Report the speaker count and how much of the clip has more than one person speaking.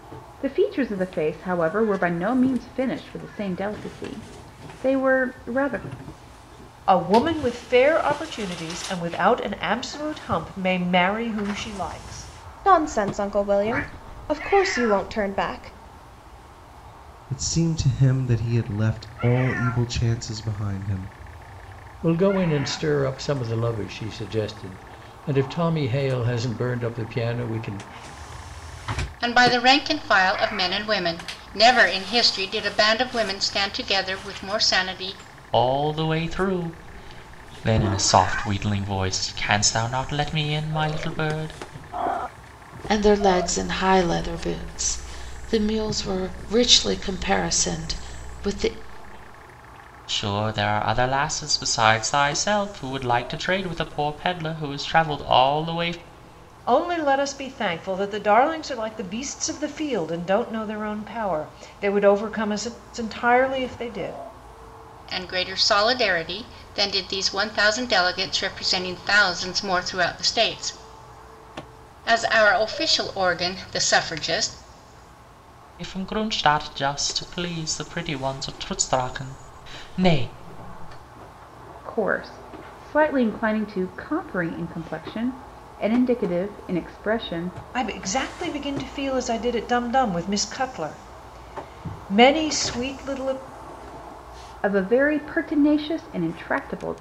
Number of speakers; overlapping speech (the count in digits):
8, no overlap